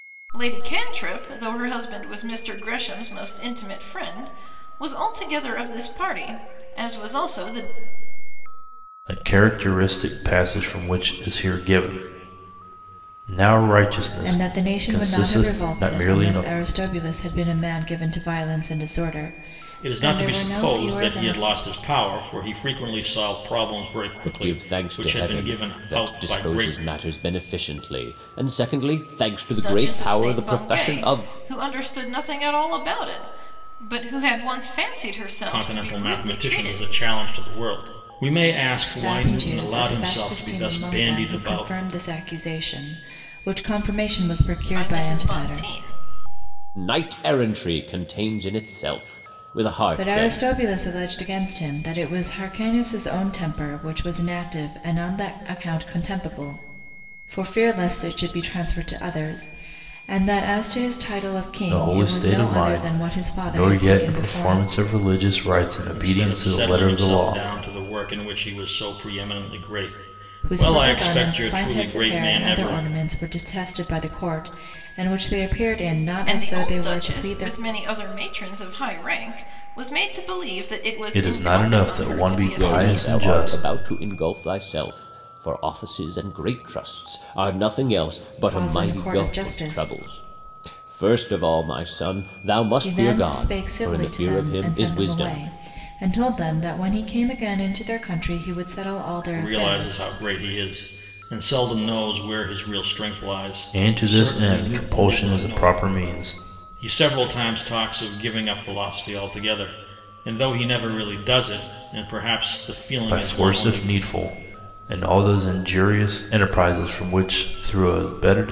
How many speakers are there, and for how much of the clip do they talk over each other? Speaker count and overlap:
5, about 28%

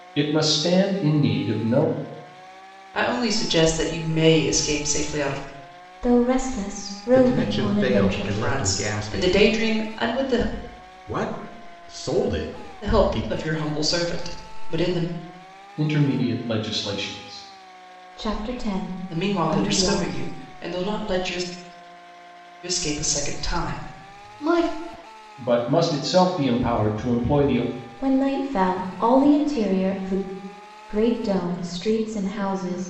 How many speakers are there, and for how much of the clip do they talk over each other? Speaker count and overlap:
4, about 12%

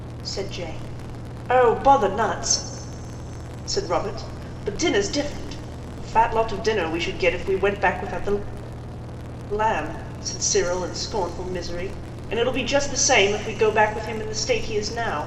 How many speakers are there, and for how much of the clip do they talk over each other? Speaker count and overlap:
1, no overlap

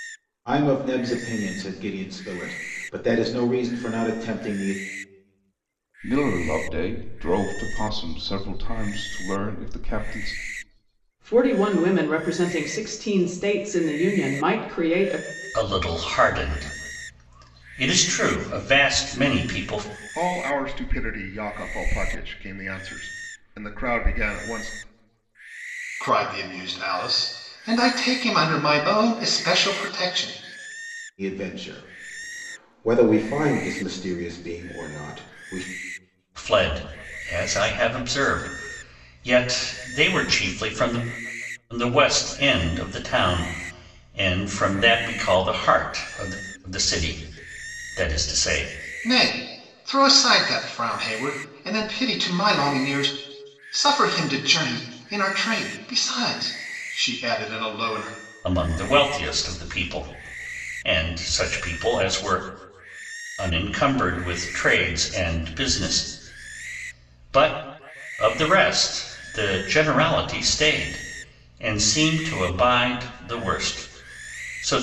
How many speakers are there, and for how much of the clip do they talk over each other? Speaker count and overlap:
6, no overlap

